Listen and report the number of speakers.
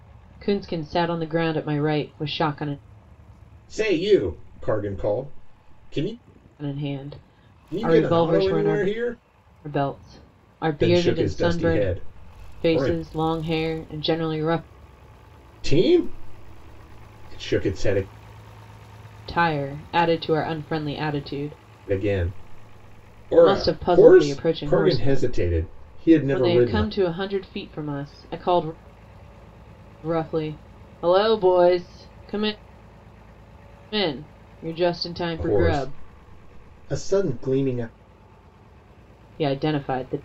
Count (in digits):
2